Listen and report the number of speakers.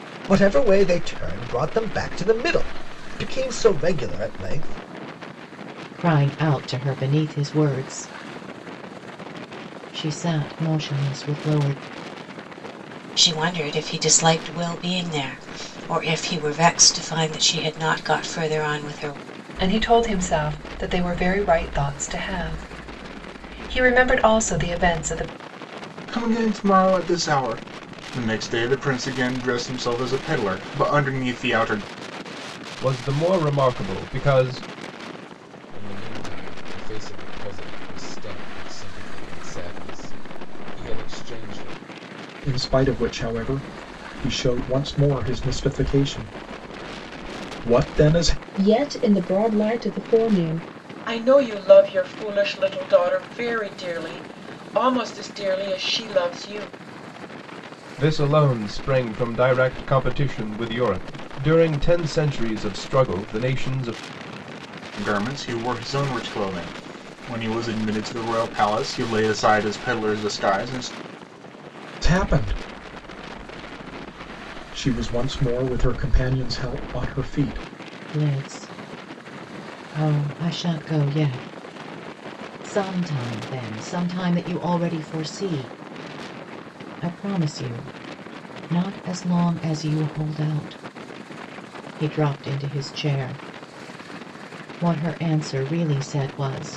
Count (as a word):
ten